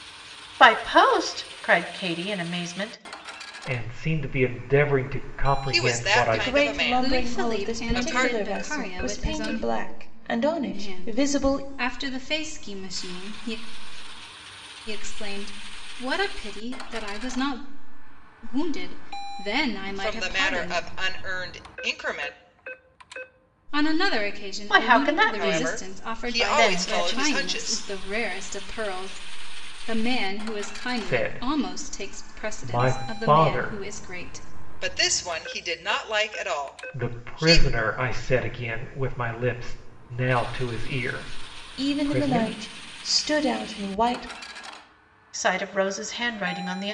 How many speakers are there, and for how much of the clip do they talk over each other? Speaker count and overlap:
5, about 29%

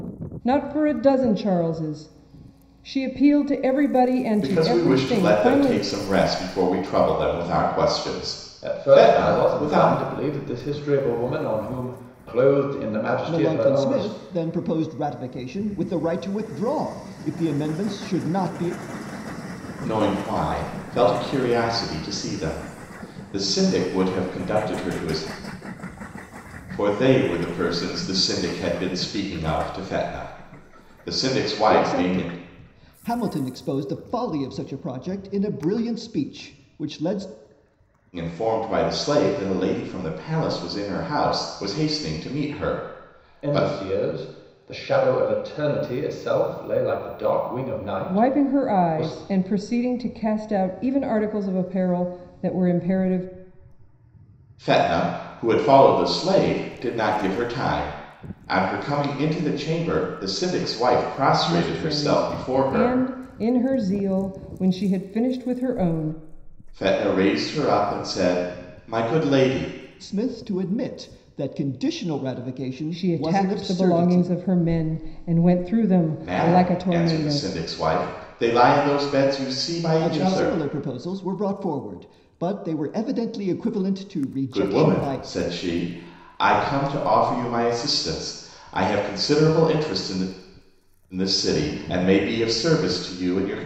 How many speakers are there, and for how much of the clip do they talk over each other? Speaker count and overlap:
4, about 12%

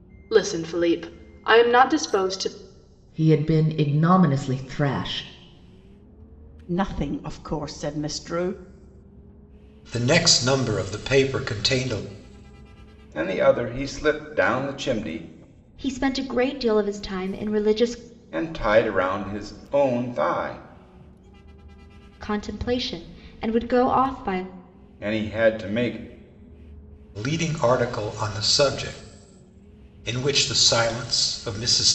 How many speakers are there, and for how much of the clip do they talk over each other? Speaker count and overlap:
6, no overlap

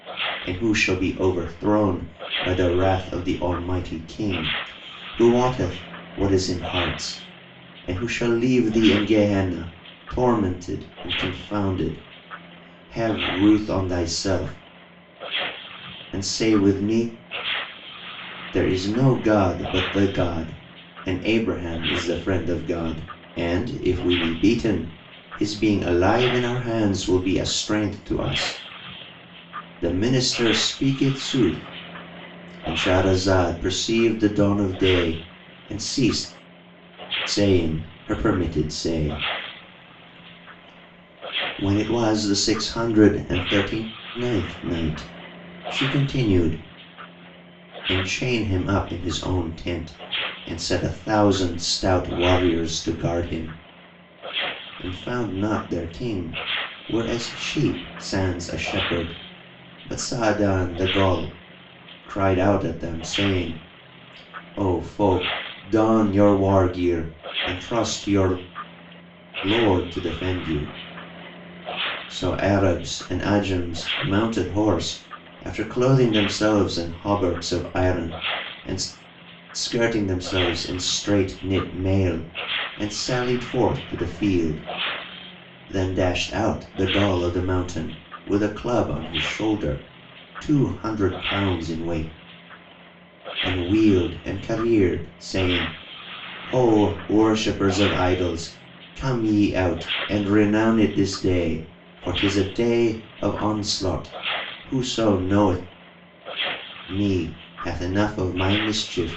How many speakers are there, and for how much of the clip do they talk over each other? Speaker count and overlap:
1, no overlap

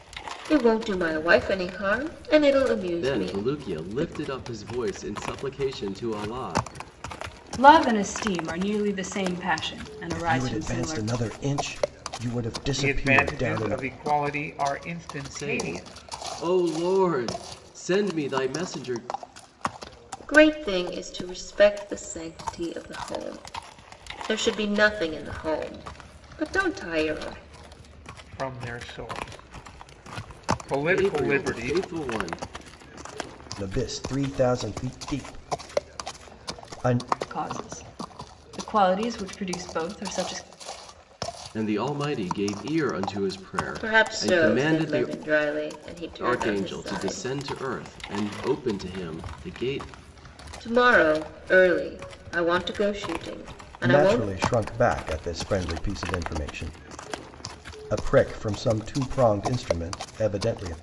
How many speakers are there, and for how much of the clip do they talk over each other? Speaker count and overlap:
5, about 13%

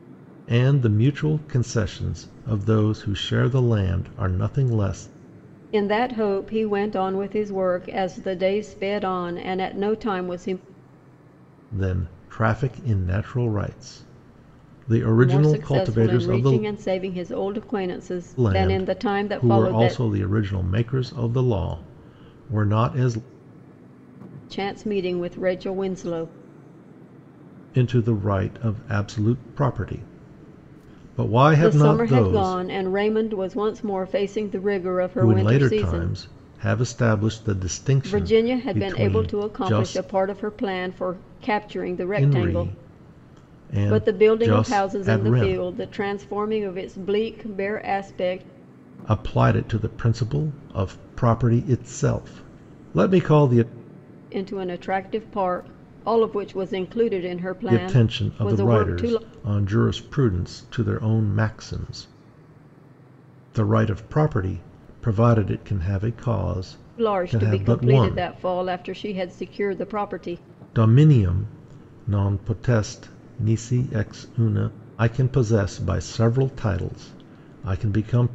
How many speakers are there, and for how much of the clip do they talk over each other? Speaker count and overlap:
2, about 16%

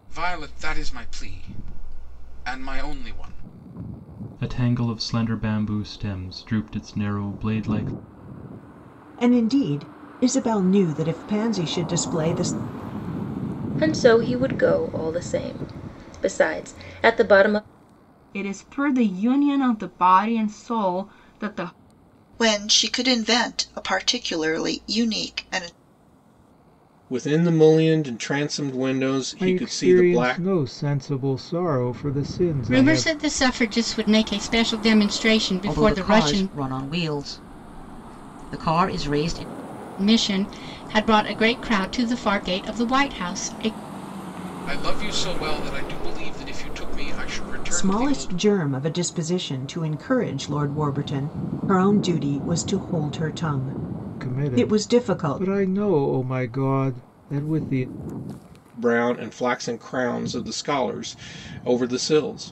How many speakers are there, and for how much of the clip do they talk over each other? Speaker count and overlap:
10, about 7%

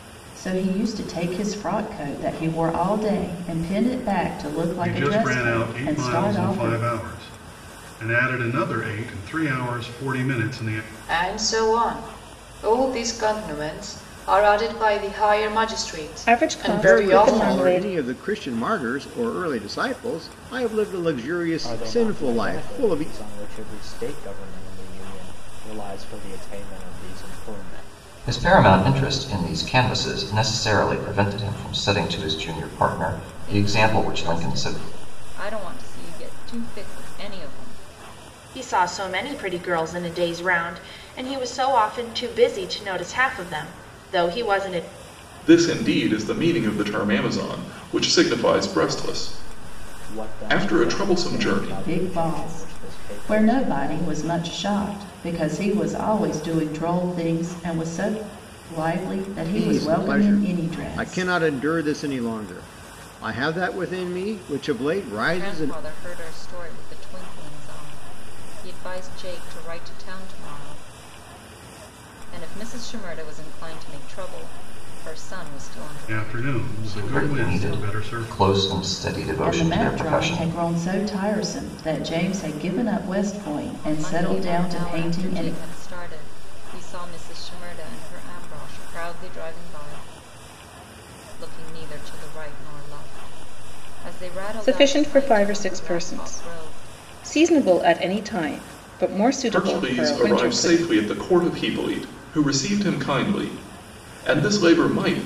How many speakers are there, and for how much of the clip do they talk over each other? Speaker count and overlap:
10, about 22%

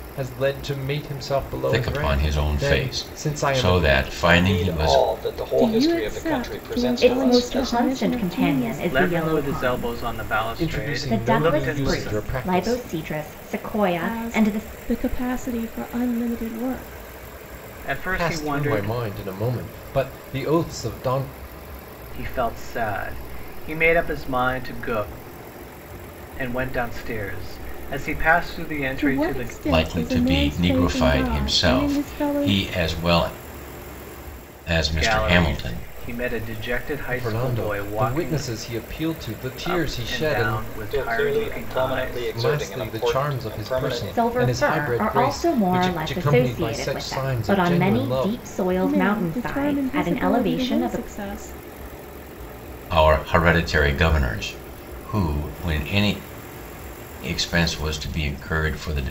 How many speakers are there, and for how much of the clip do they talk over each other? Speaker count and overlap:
6, about 47%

